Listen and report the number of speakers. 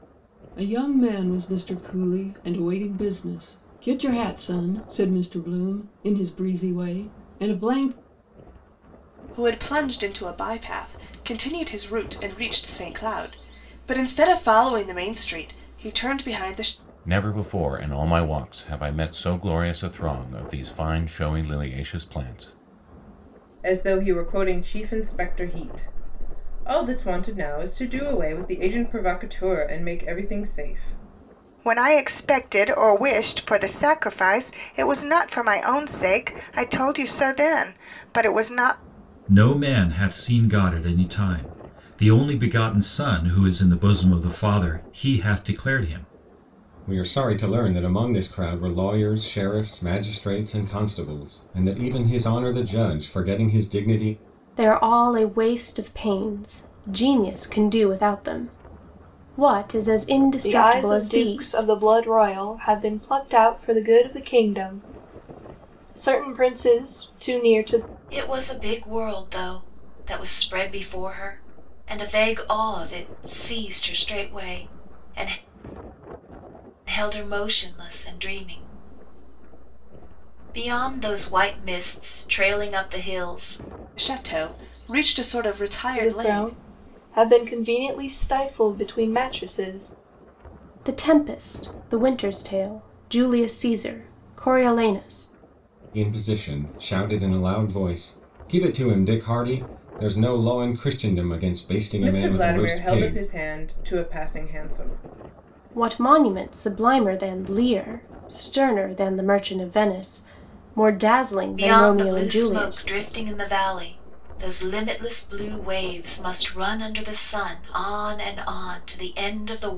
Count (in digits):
10